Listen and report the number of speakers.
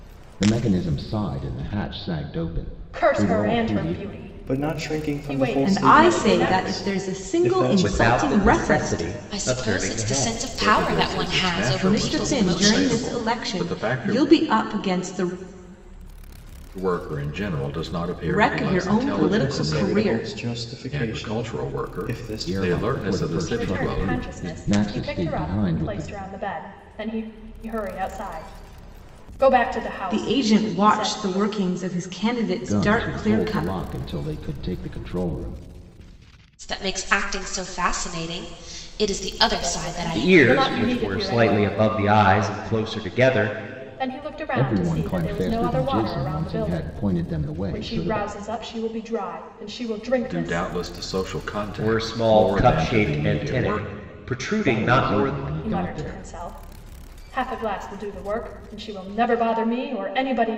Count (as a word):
seven